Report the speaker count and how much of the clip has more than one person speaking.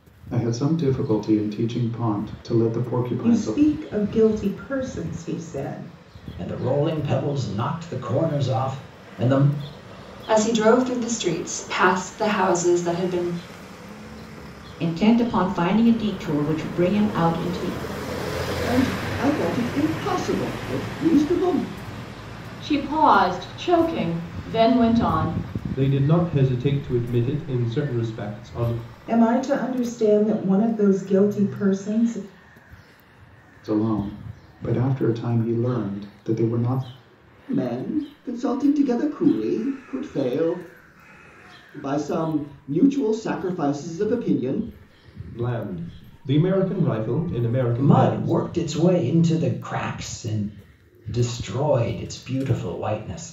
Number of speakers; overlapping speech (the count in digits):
8, about 2%